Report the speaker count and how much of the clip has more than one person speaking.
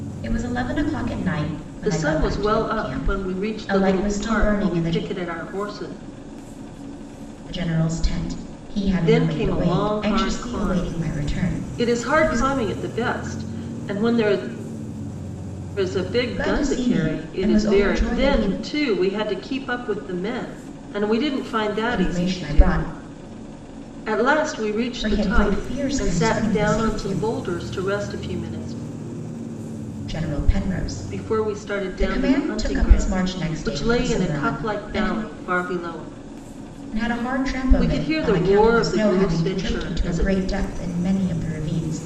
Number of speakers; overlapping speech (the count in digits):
2, about 42%